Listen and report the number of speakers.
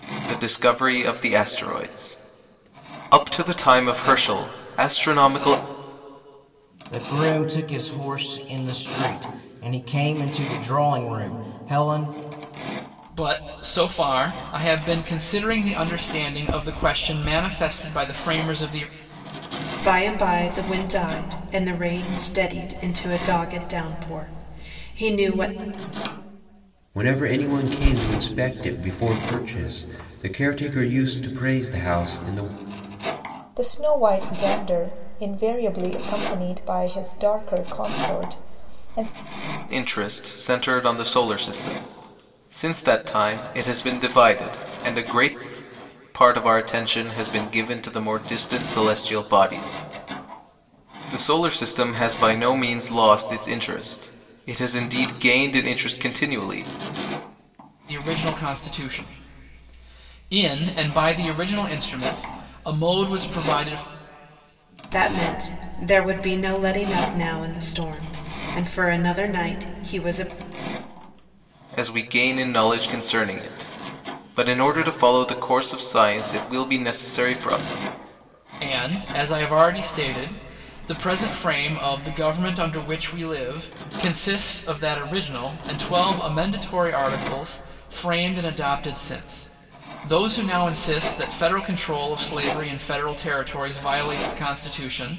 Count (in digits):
6